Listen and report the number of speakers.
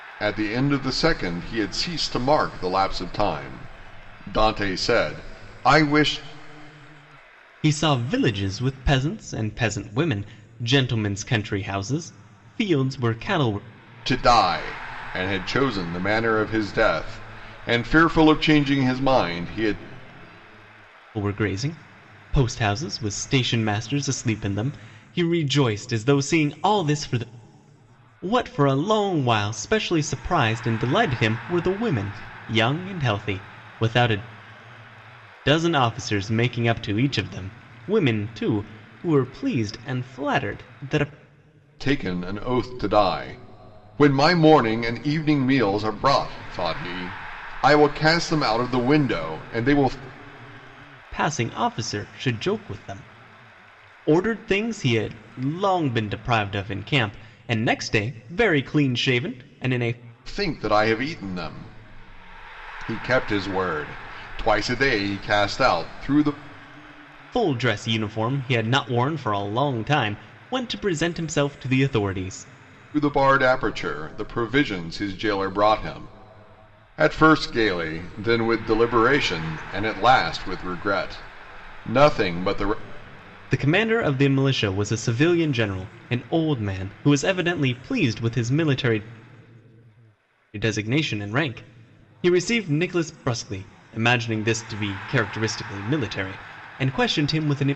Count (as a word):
two